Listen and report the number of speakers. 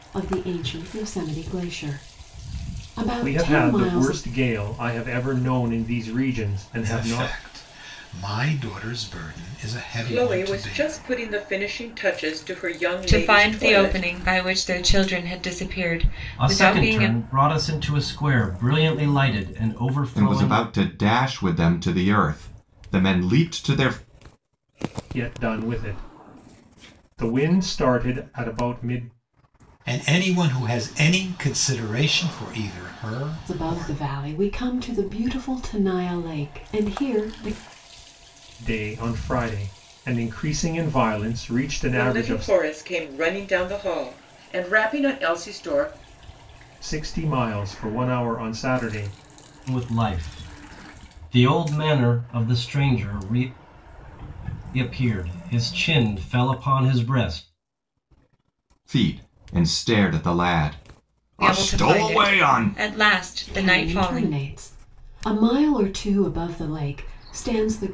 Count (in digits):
7